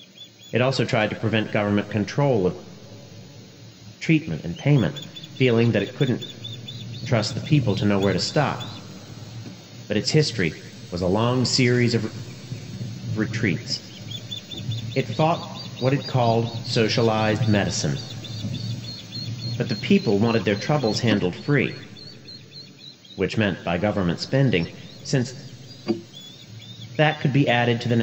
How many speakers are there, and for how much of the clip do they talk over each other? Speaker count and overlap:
1, no overlap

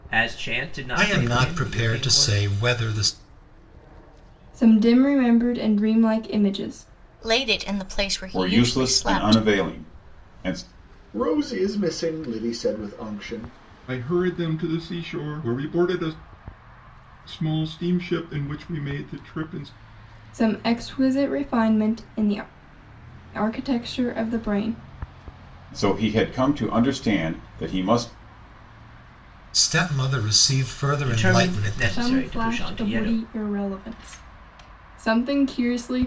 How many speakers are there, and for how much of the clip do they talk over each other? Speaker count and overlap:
7, about 14%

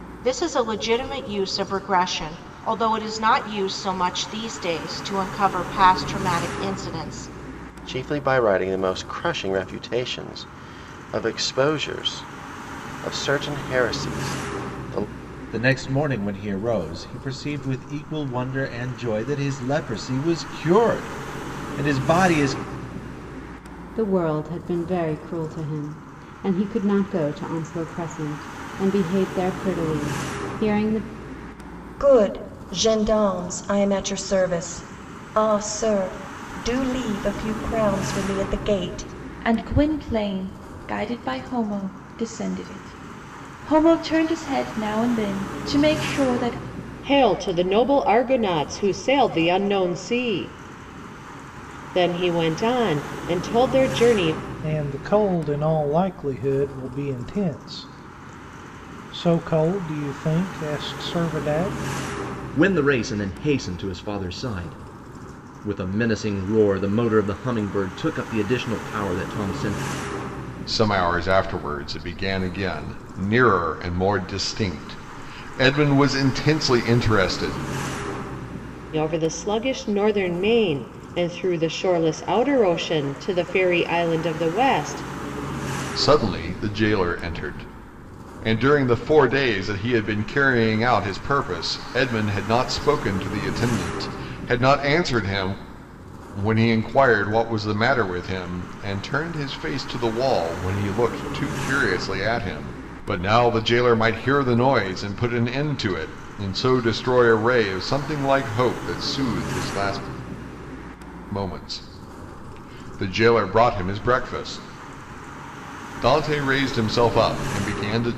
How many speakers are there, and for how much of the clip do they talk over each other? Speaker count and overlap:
10, no overlap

